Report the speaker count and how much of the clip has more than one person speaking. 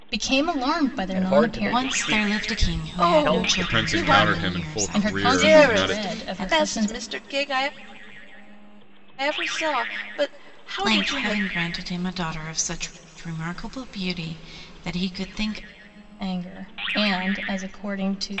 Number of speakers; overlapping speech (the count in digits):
5, about 36%